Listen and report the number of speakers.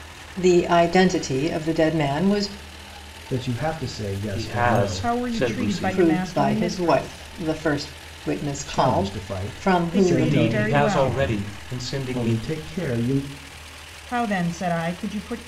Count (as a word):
four